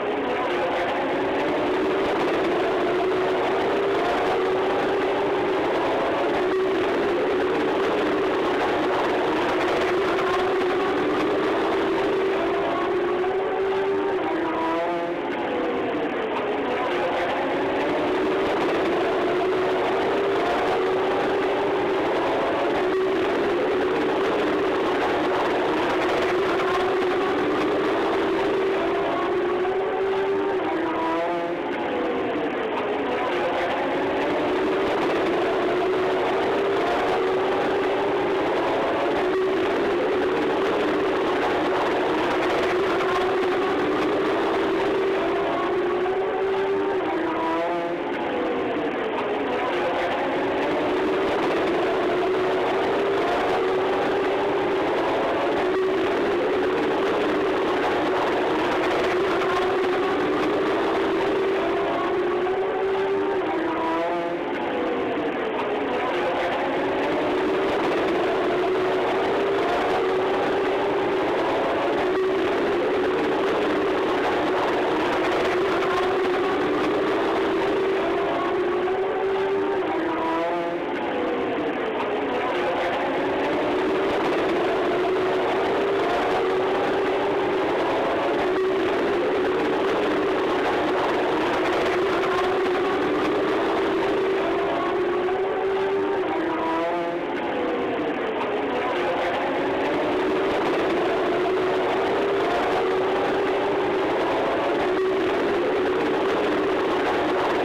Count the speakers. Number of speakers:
zero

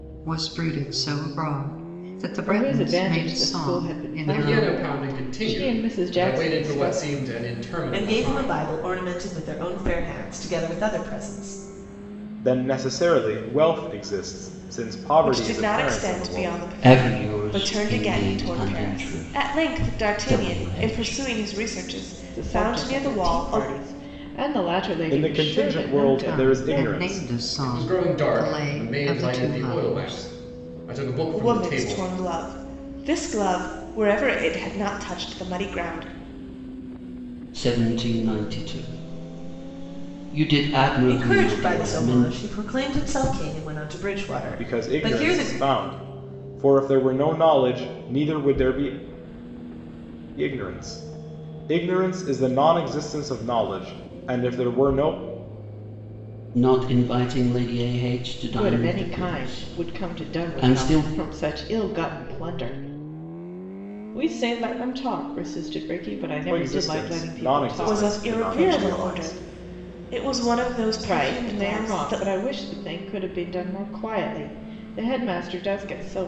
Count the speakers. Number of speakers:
seven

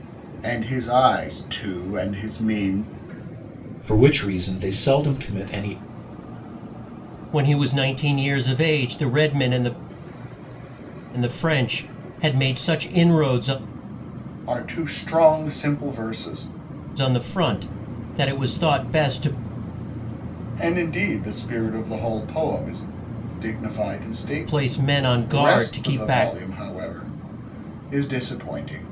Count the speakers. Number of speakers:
three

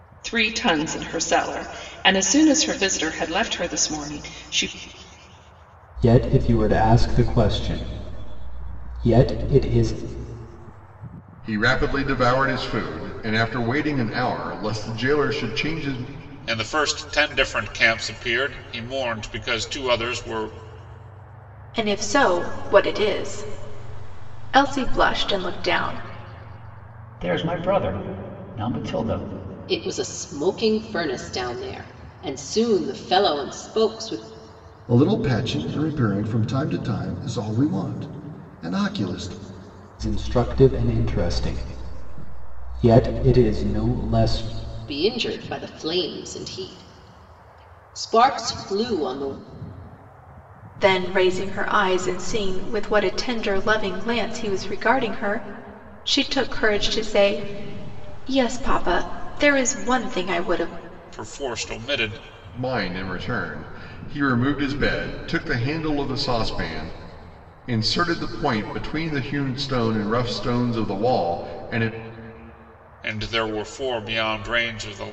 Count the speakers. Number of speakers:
eight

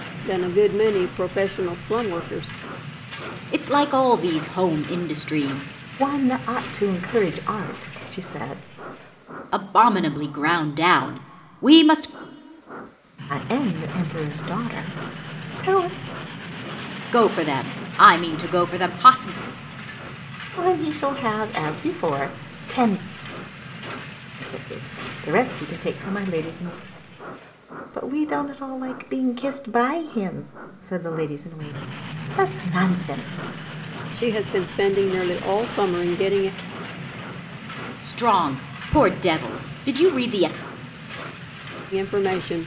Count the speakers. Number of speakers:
three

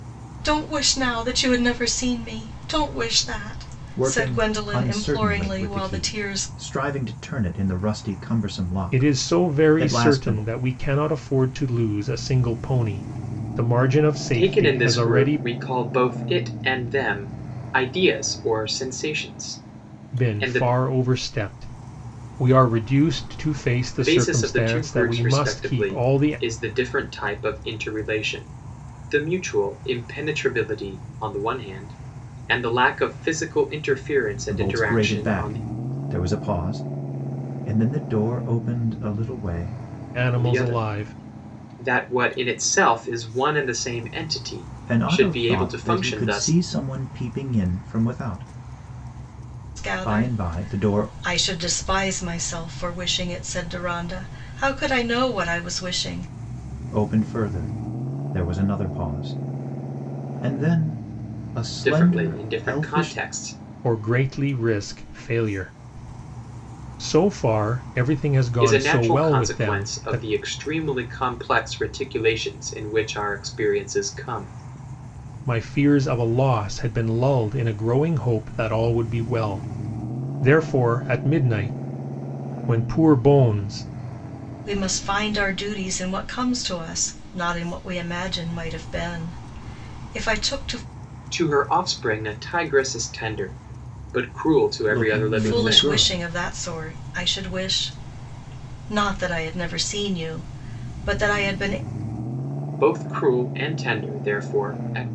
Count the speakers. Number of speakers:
four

